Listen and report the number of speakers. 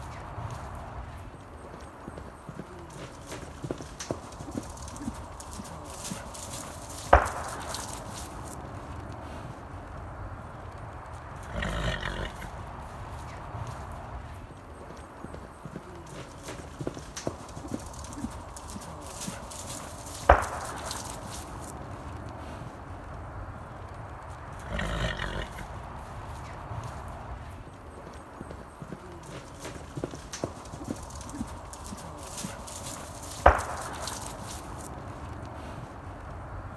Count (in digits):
0